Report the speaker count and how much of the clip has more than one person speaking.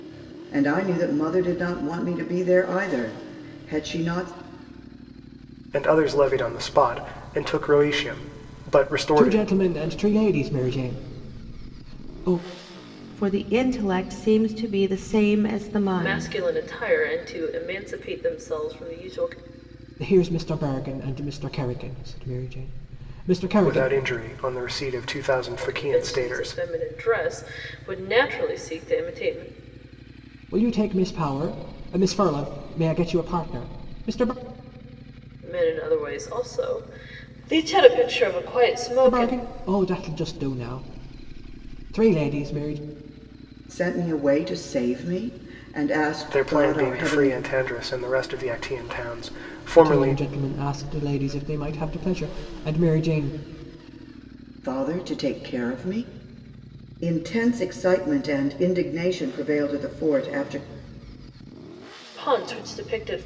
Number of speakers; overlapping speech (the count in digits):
5, about 6%